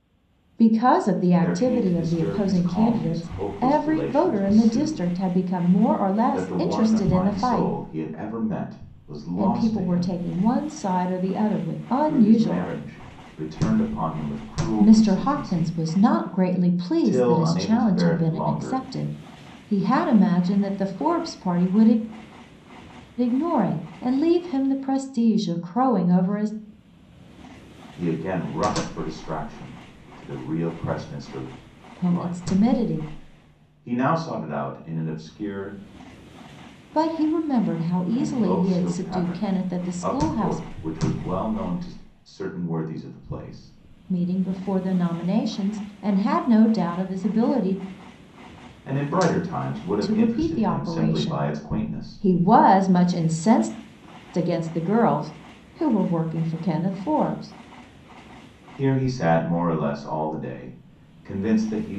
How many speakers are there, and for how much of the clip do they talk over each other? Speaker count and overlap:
2, about 25%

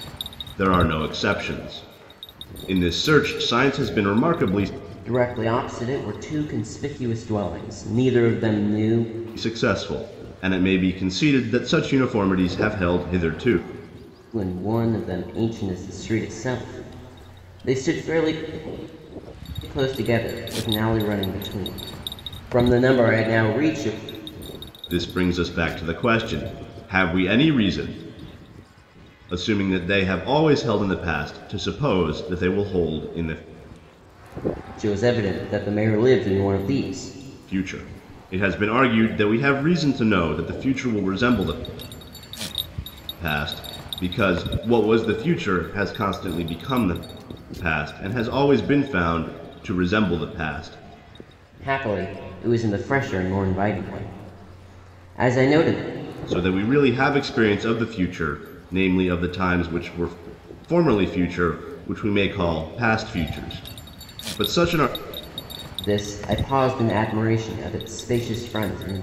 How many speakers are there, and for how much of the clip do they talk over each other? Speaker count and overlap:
2, no overlap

